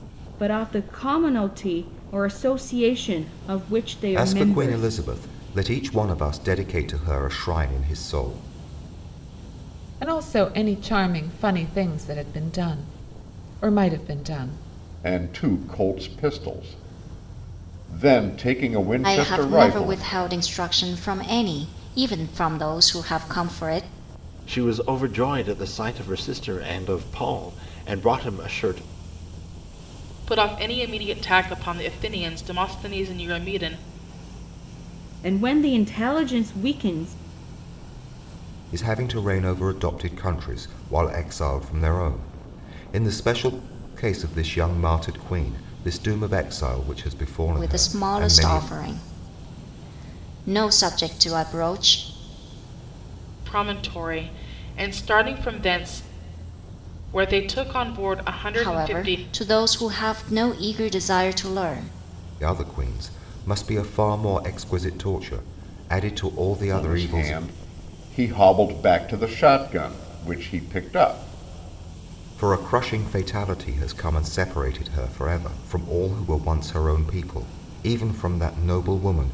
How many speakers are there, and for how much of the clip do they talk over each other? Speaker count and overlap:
7, about 5%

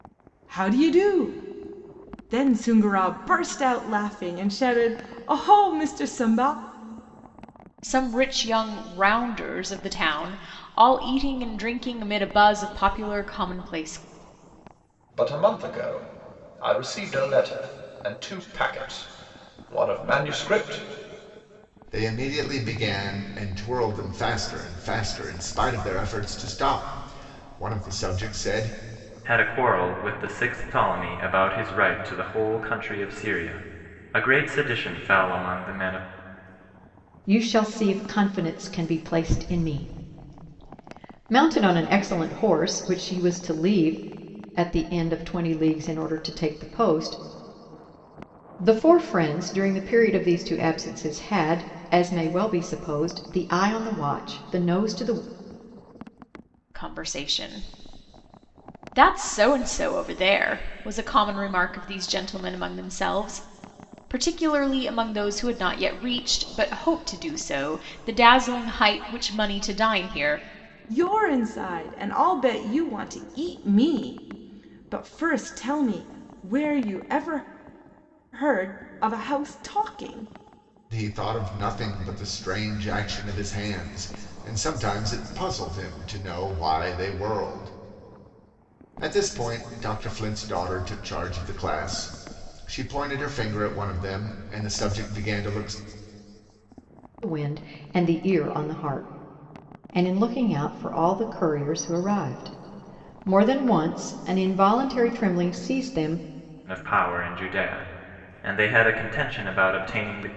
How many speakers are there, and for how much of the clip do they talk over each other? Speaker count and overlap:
6, no overlap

